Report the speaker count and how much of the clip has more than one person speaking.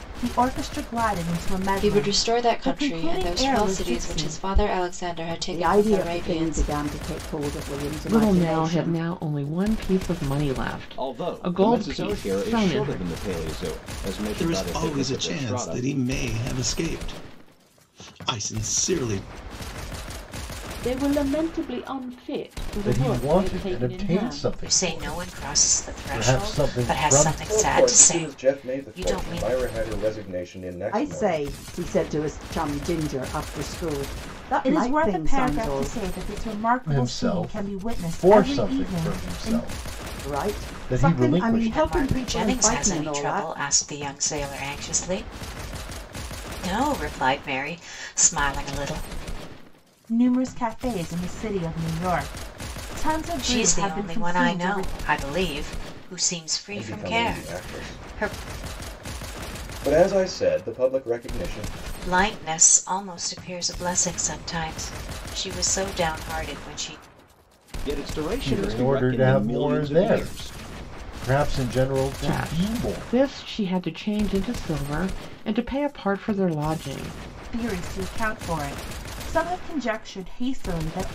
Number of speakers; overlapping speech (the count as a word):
ten, about 37%